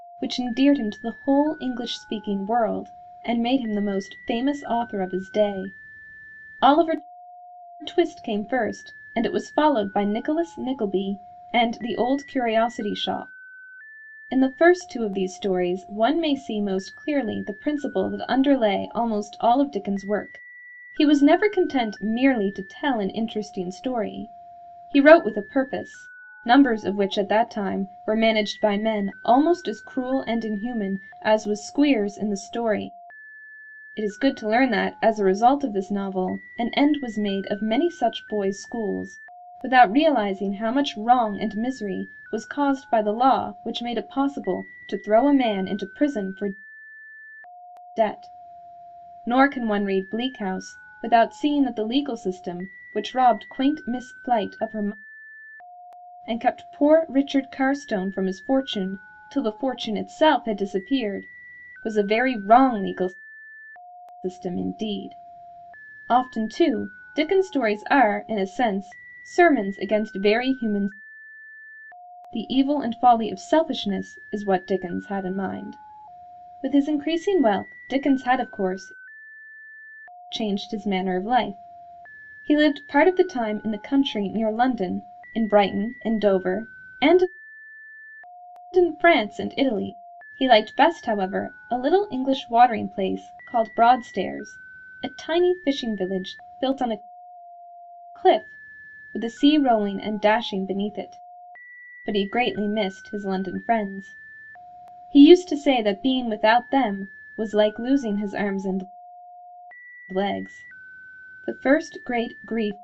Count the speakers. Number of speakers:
1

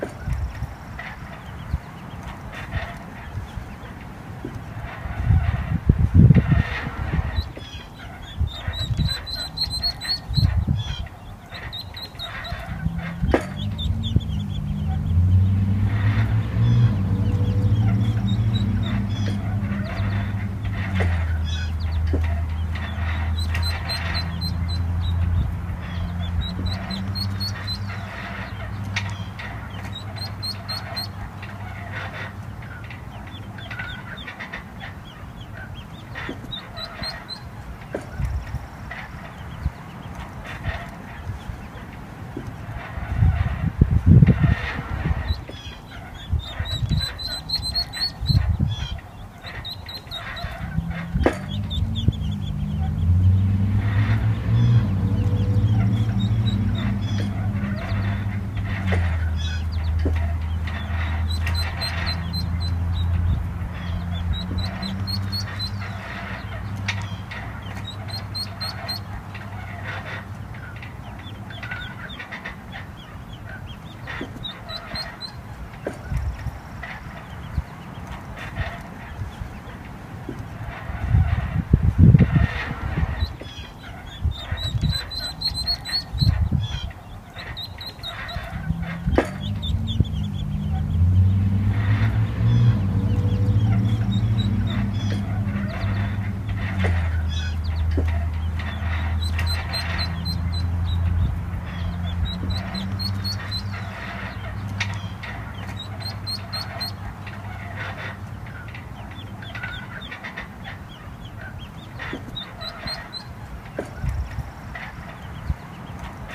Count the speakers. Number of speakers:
0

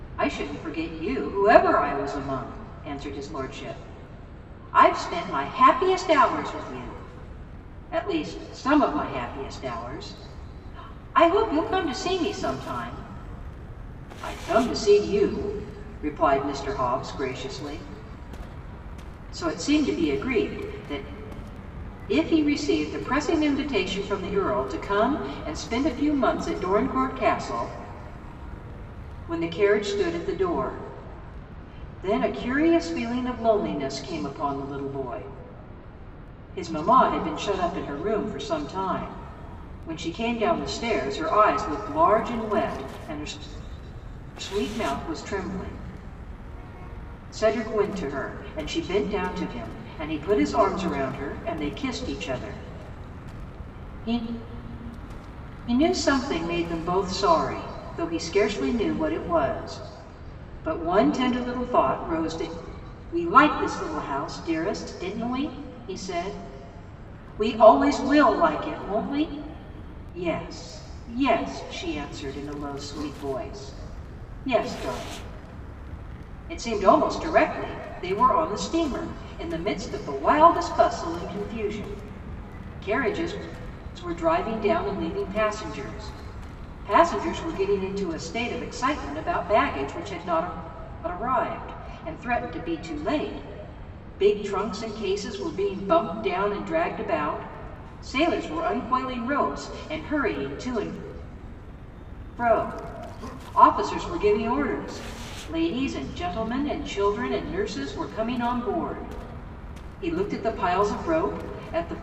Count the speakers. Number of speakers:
1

